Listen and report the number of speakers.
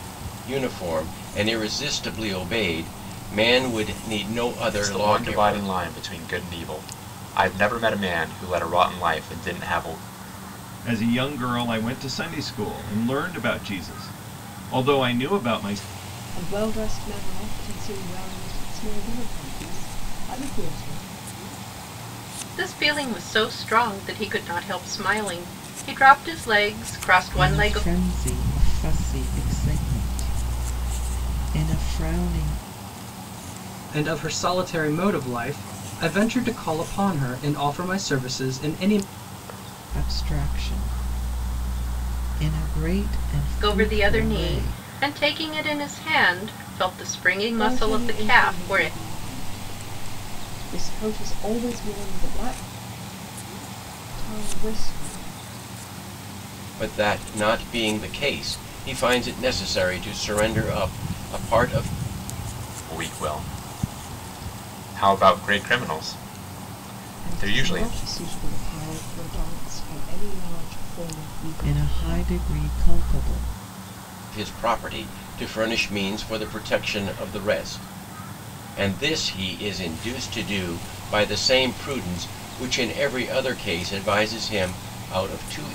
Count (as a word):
seven